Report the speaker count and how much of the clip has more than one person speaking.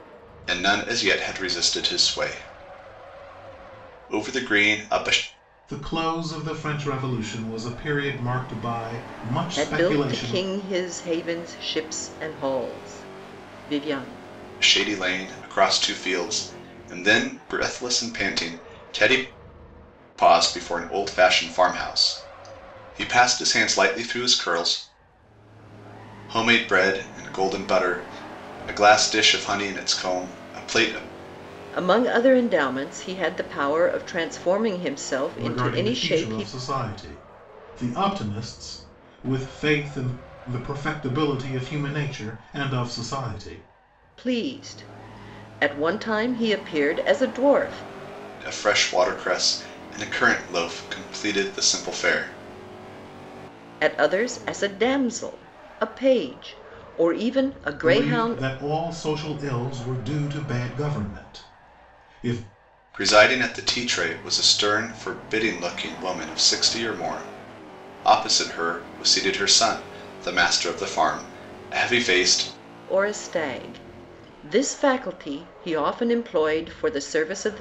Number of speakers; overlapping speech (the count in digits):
3, about 4%